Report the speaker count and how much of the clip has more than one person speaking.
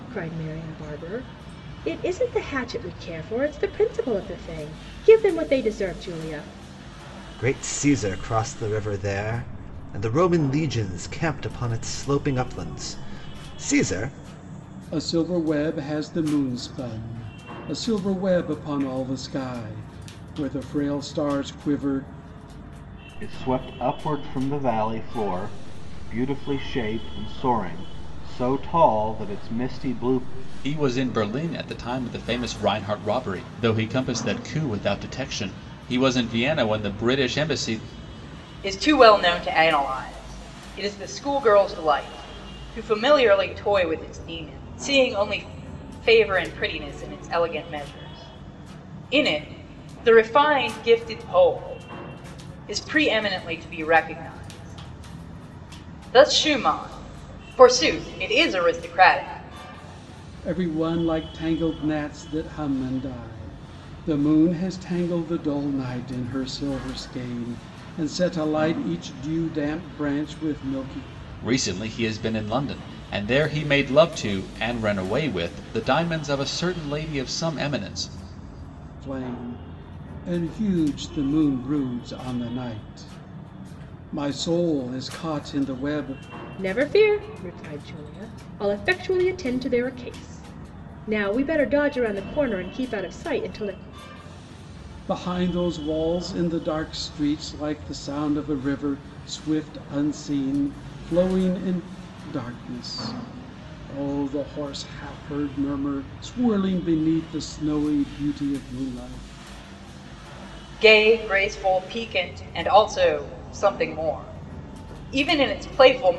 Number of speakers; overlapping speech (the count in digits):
6, no overlap